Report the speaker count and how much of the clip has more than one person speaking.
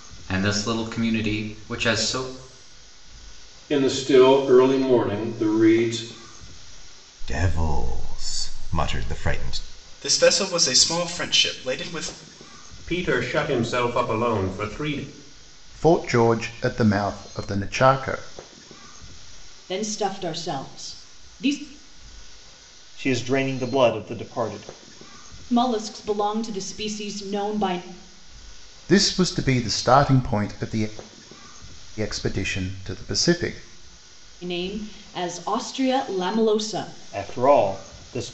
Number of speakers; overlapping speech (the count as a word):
eight, no overlap